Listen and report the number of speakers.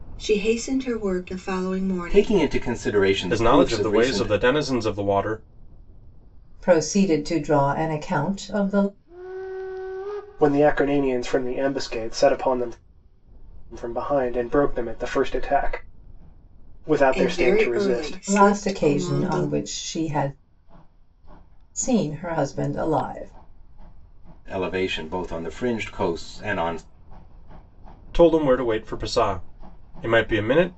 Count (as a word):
five